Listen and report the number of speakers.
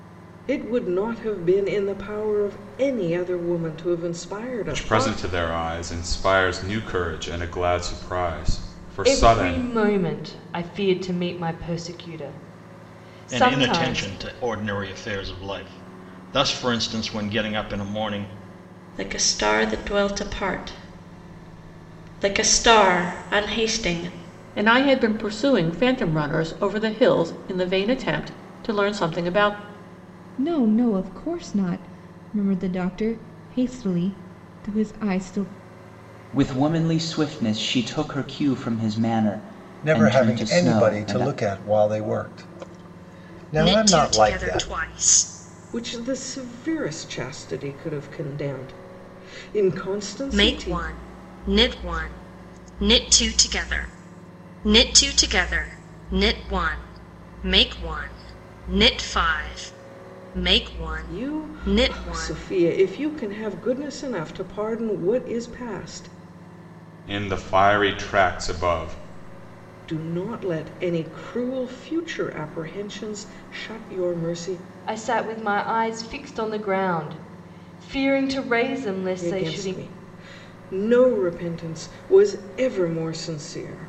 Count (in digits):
10